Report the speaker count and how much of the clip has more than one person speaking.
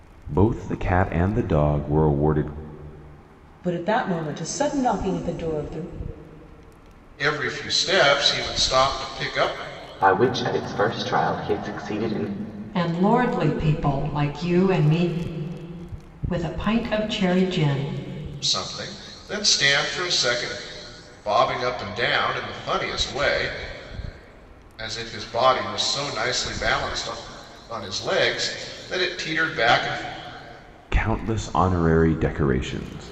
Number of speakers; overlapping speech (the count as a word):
five, no overlap